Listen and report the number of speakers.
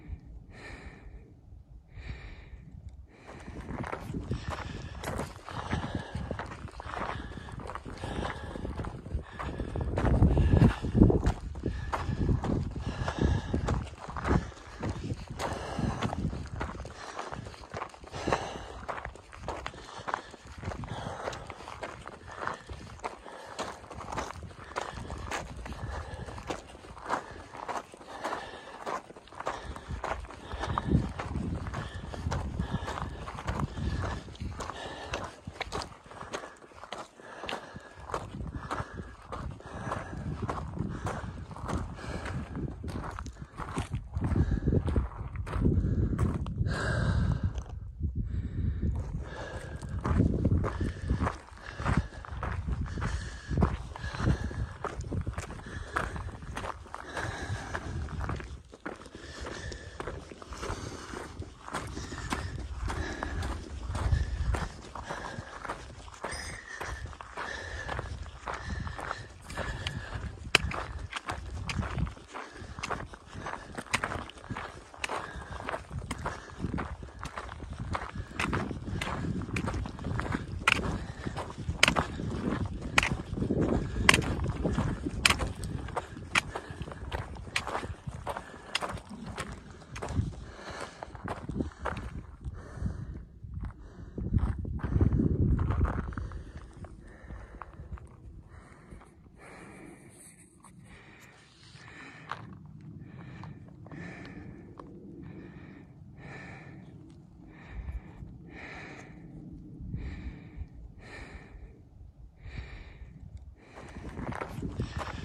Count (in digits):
0